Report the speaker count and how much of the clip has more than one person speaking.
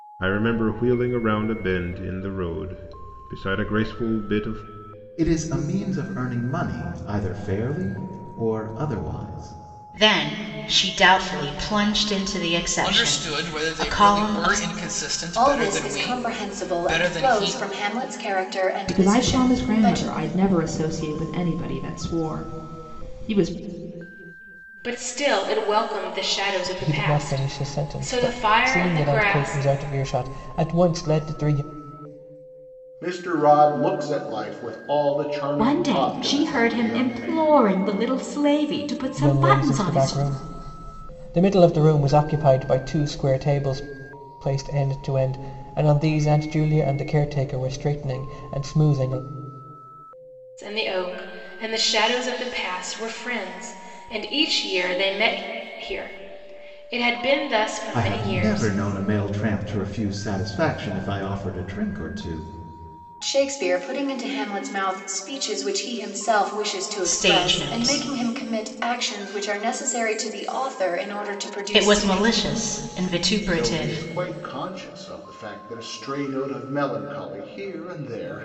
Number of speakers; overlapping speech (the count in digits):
10, about 18%